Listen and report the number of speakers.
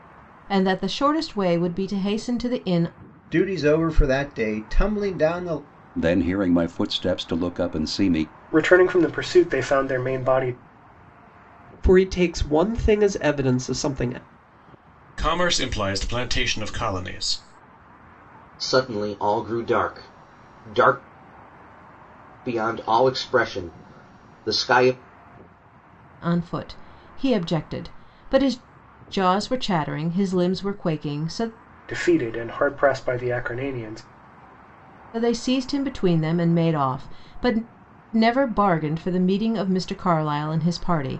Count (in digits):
7